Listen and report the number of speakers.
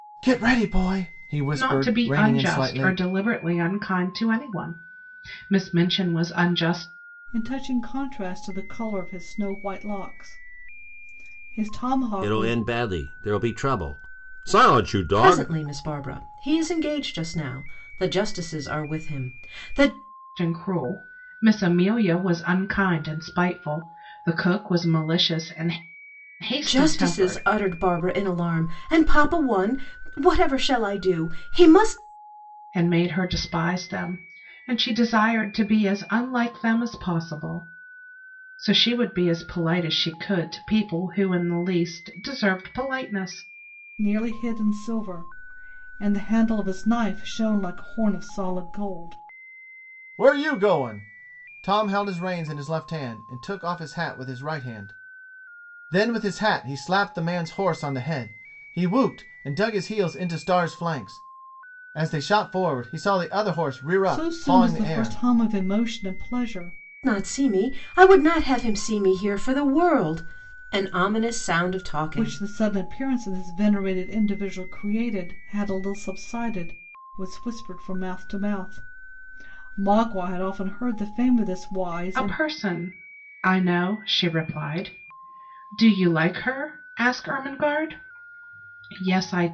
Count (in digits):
5